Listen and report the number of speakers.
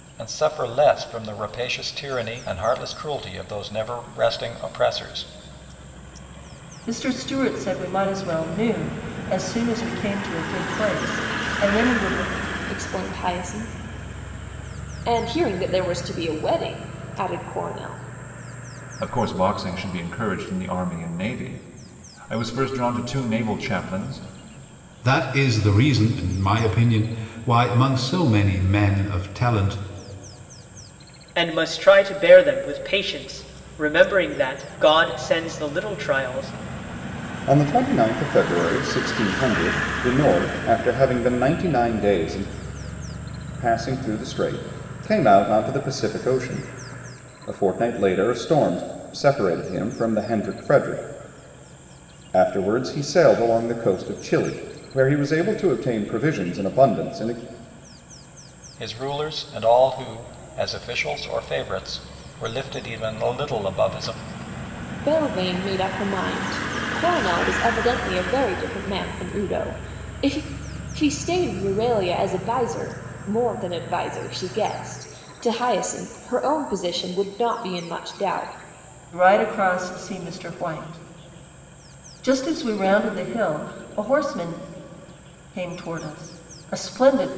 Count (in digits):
7